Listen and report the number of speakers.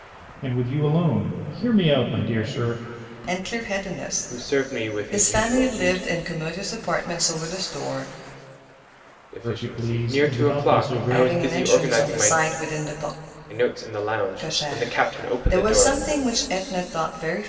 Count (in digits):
3